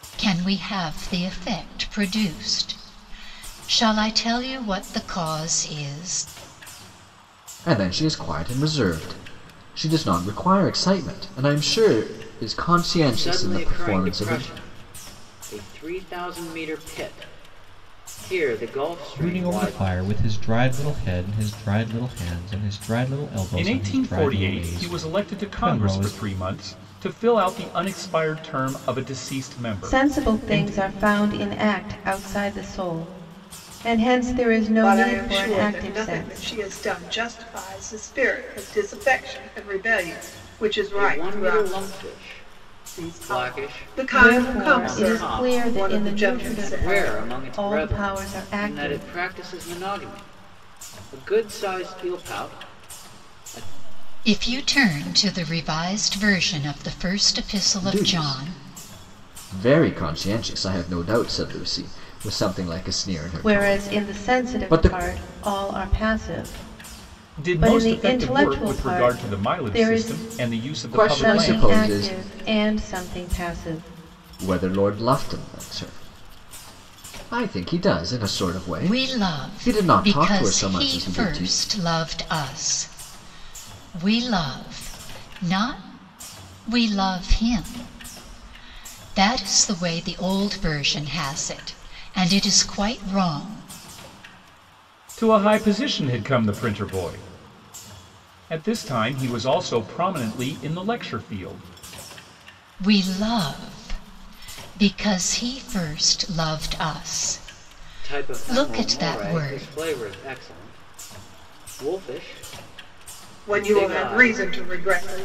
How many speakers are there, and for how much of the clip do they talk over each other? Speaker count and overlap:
seven, about 23%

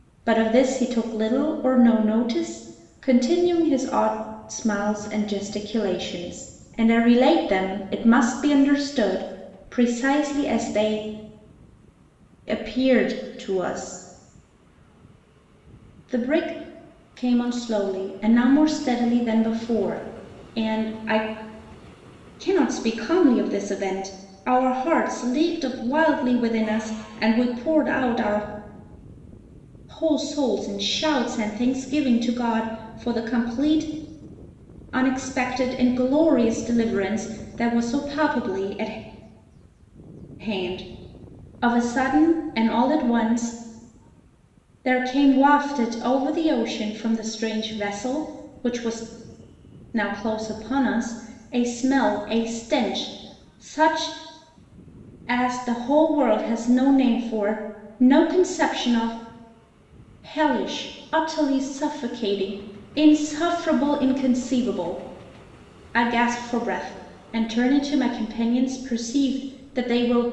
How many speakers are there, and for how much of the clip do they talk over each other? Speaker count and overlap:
one, no overlap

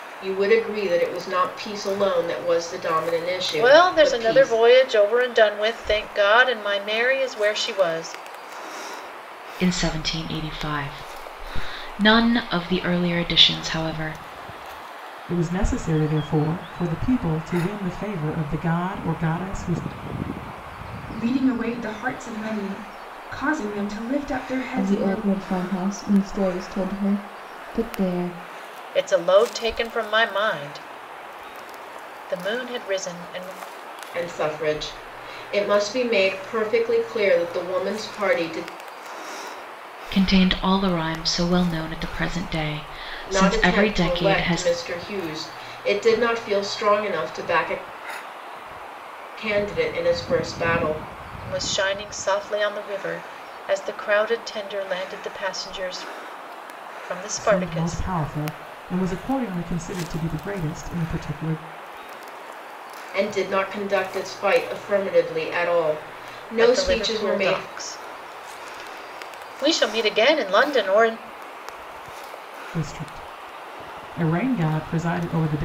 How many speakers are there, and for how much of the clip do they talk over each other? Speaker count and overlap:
six, about 6%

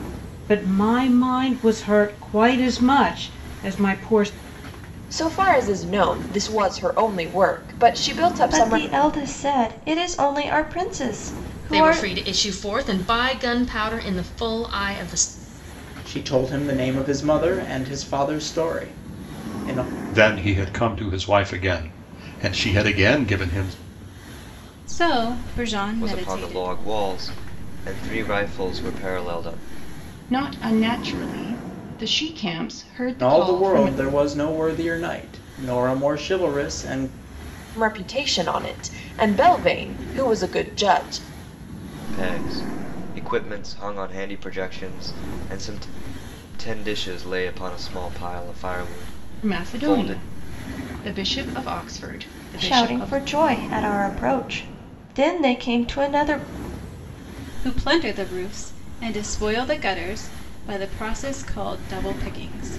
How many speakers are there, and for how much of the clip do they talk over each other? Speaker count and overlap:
nine, about 6%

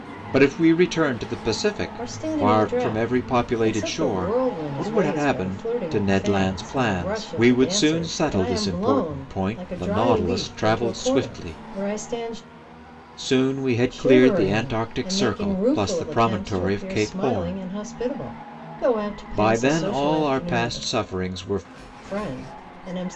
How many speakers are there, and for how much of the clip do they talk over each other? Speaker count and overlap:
two, about 65%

